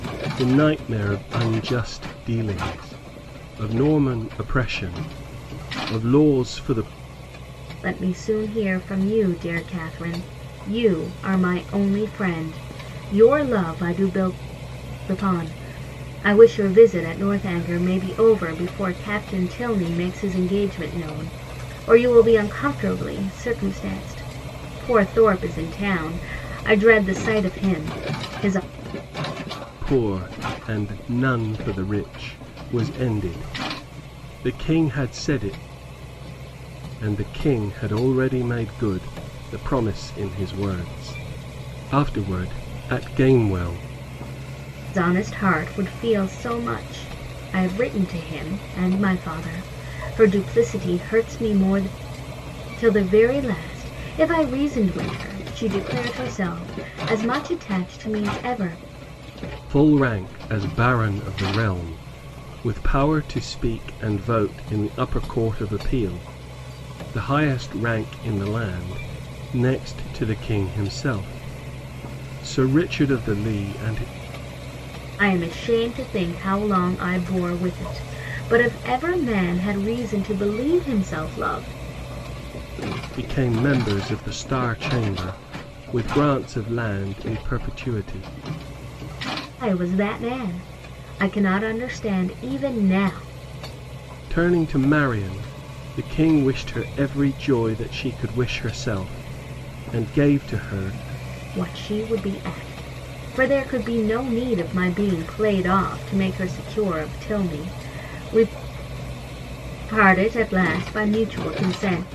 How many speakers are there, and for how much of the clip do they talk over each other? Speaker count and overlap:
2, no overlap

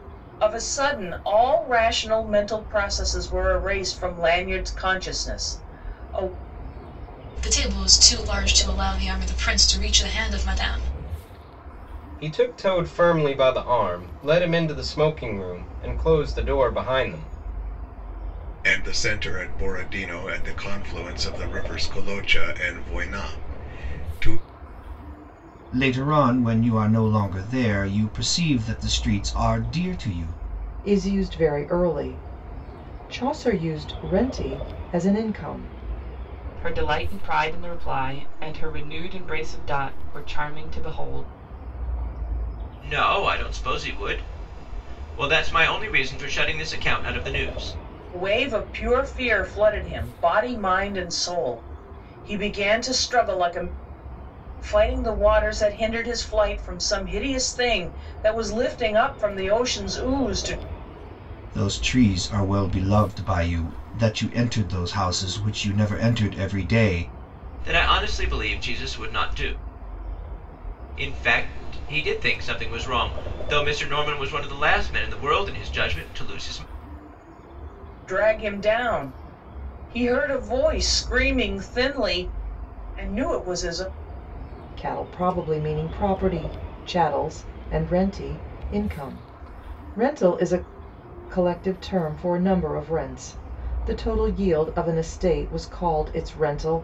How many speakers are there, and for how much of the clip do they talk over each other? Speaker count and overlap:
8, no overlap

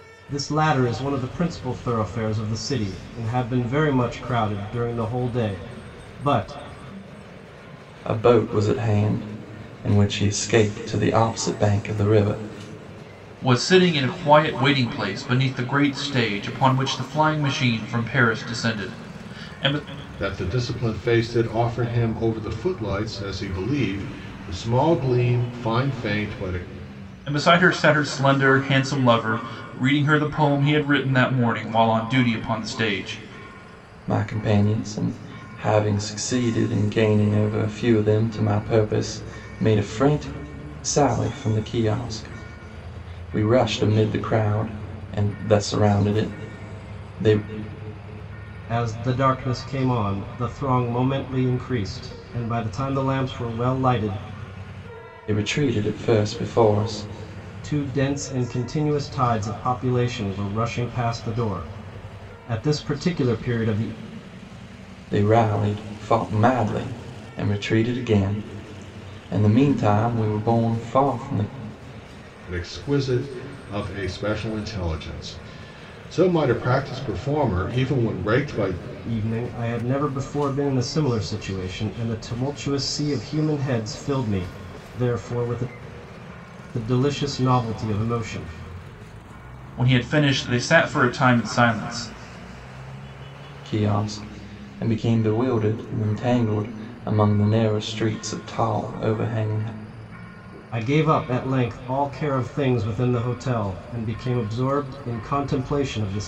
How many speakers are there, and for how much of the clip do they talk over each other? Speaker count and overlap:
4, no overlap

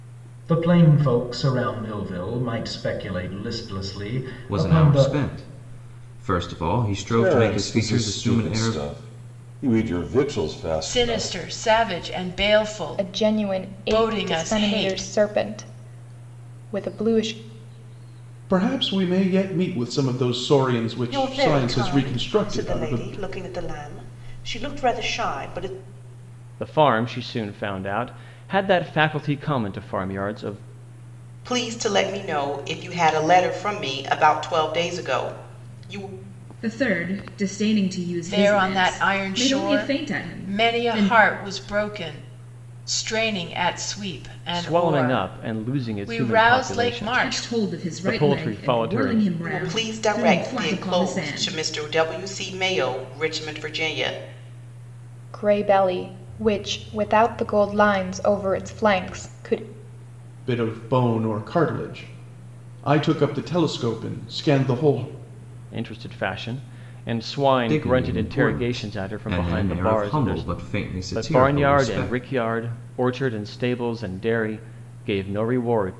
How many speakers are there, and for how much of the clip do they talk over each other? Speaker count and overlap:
10, about 28%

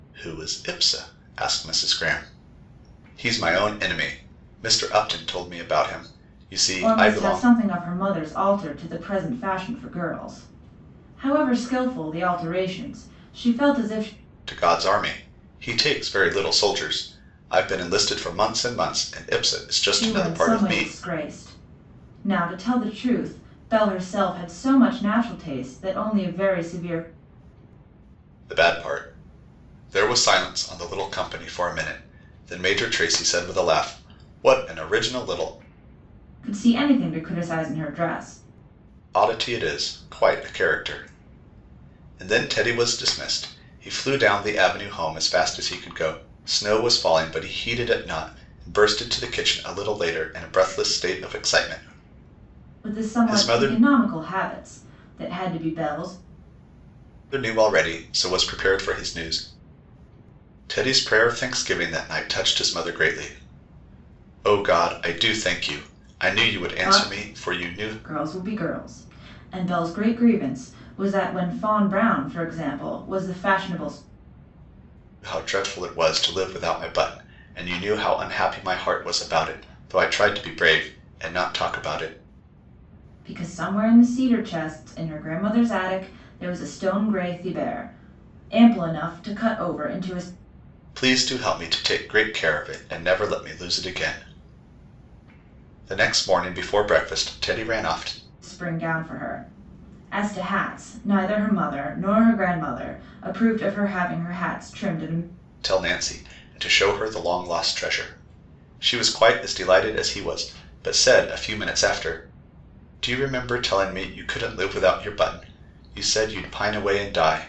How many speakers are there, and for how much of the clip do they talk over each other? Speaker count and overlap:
2, about 3%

